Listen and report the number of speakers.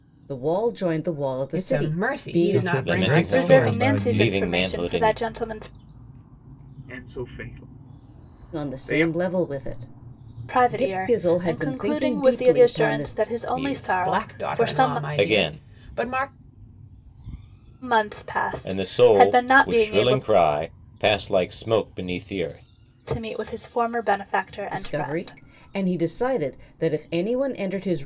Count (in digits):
6